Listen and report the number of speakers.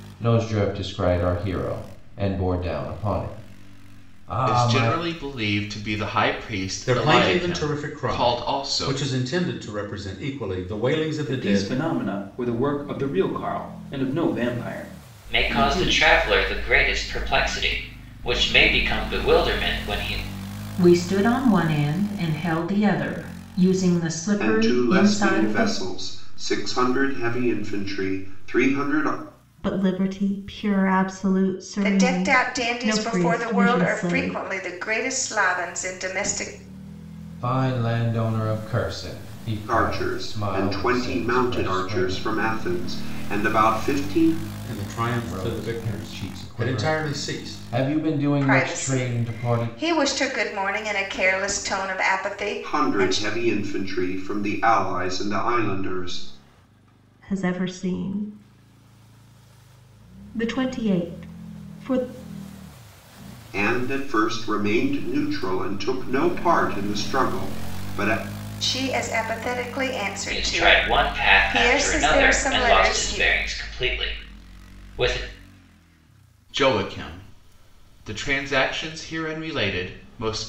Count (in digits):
9